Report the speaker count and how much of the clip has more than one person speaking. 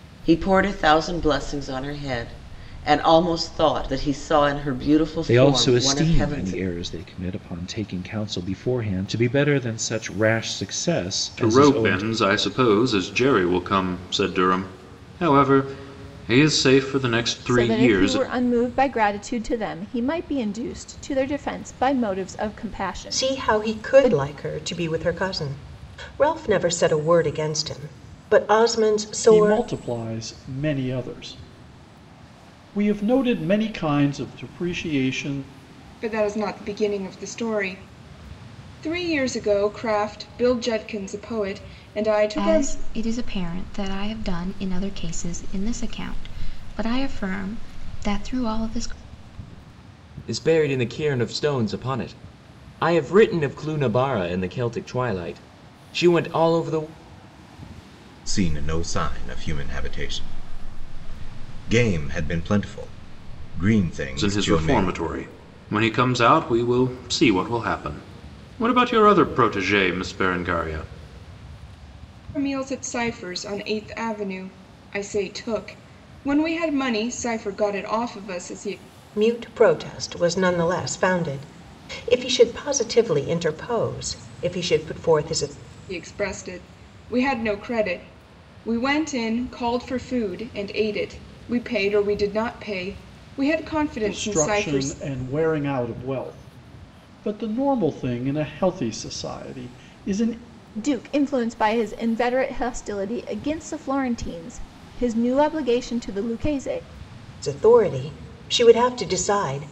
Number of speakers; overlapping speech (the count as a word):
ten, about 6%